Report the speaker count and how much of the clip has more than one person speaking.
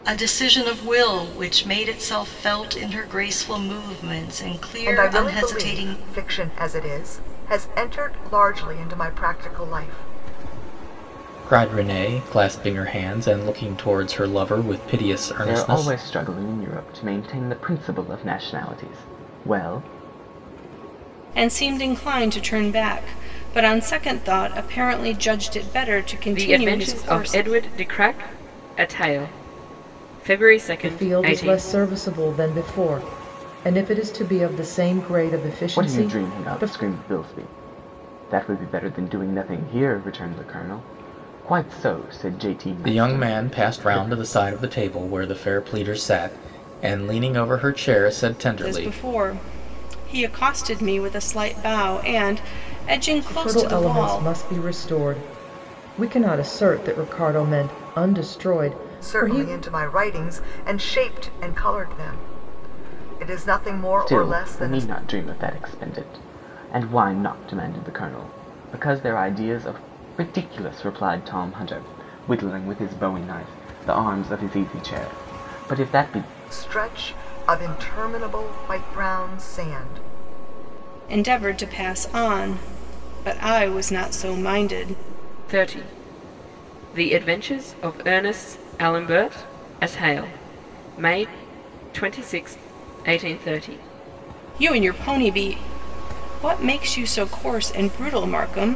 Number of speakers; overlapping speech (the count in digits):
7, about 9%